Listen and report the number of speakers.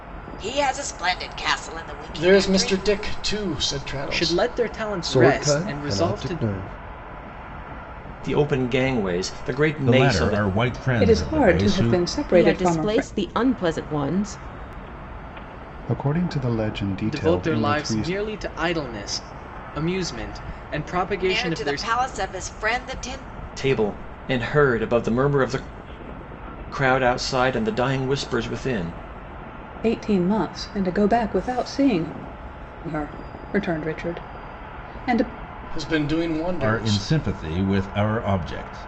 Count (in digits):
9